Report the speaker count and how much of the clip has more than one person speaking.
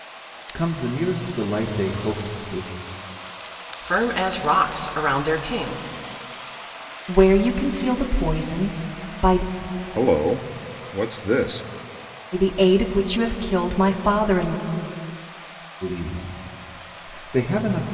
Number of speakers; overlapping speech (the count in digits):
4, no overlap